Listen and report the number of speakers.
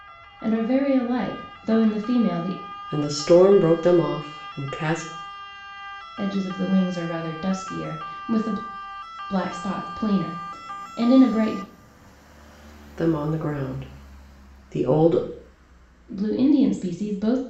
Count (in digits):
2